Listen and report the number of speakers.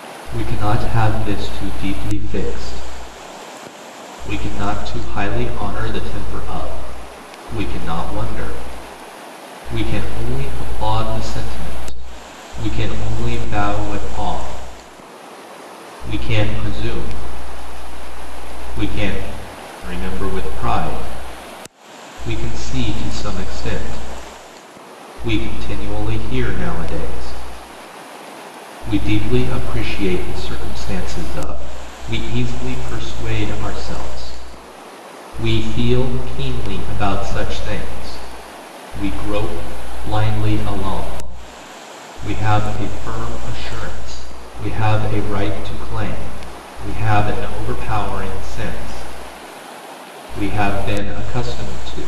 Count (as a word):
one